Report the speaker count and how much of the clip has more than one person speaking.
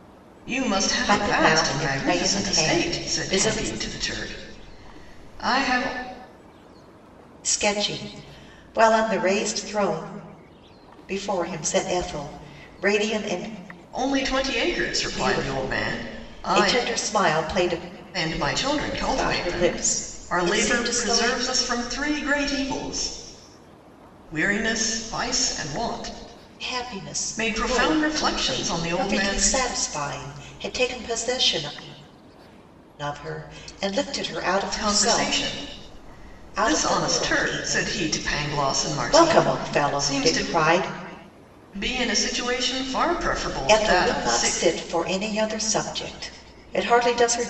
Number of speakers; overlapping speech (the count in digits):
2, about 28%